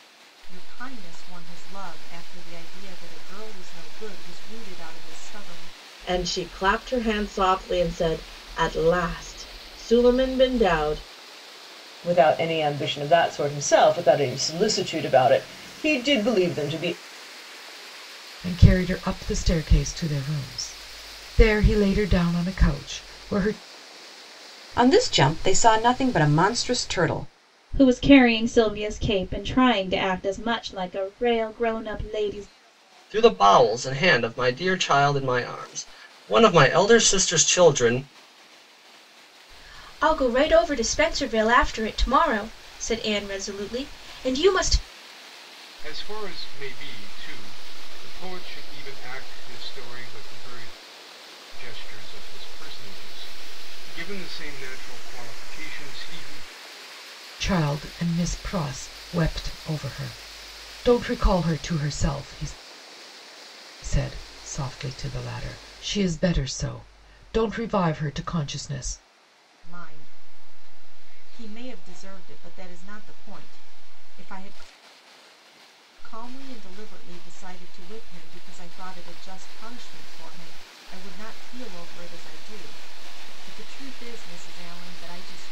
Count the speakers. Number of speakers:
9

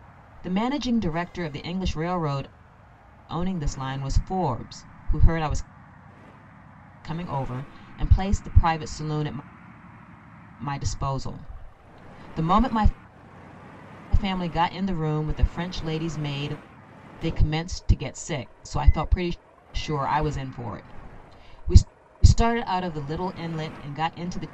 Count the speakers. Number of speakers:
1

